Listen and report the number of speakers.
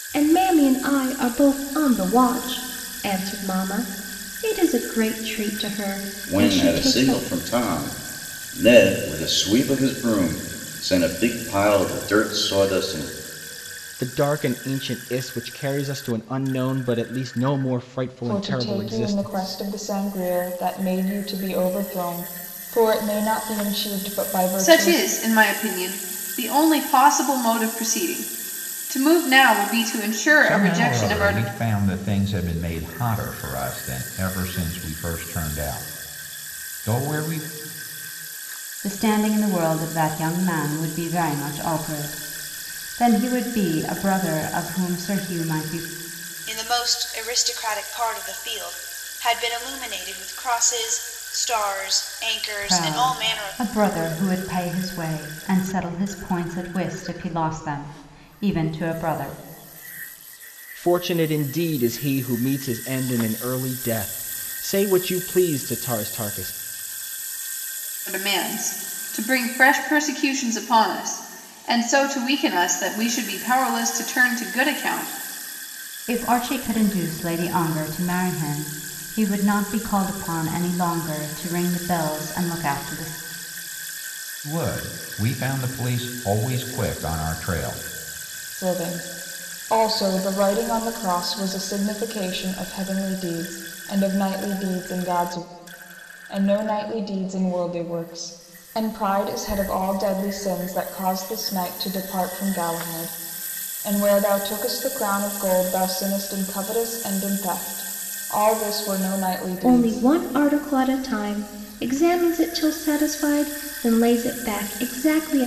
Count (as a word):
eight